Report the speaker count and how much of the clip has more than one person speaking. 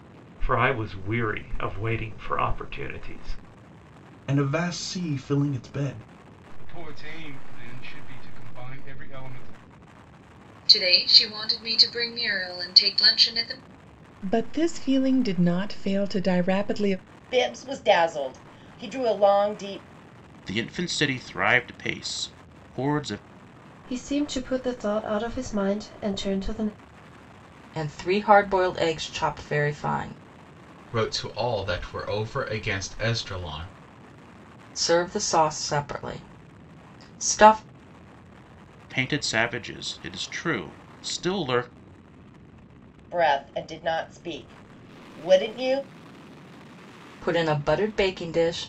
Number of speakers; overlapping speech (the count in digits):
10, no overlap